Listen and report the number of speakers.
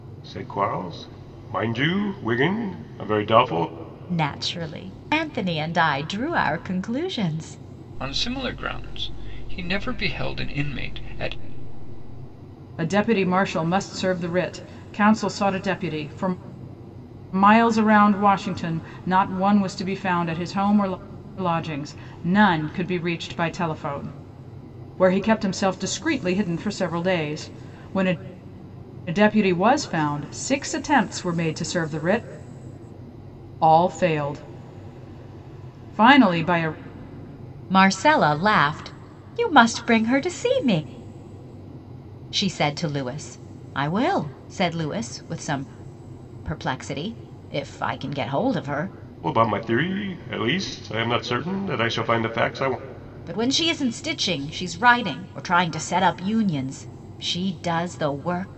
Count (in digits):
4